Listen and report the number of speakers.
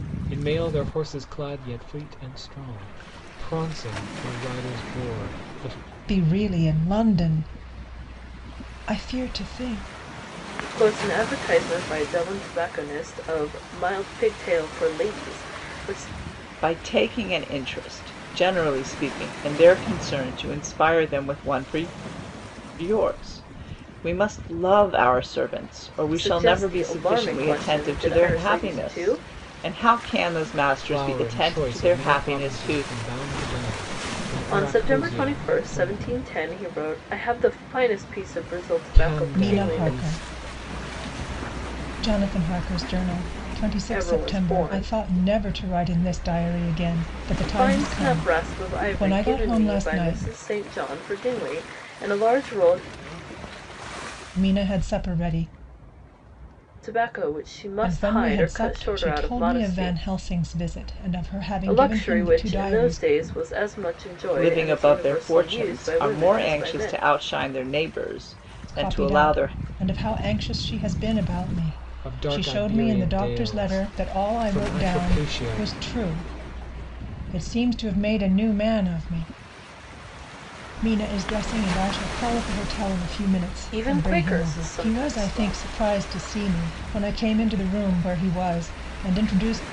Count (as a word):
four